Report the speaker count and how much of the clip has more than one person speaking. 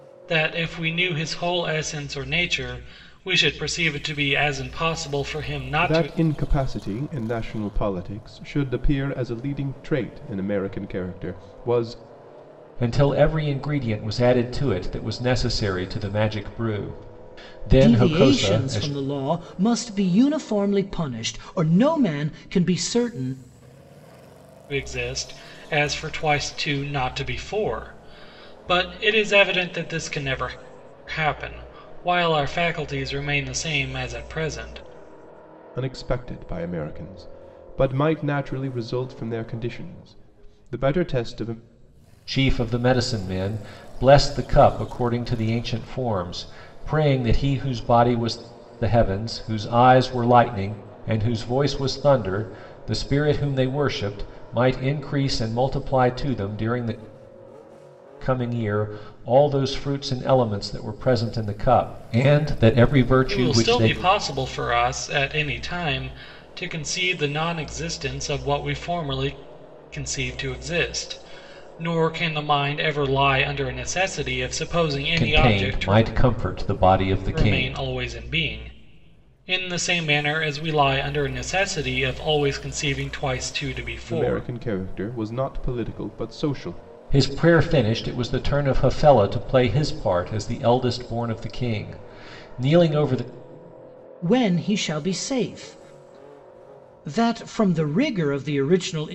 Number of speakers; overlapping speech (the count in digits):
4, about 4%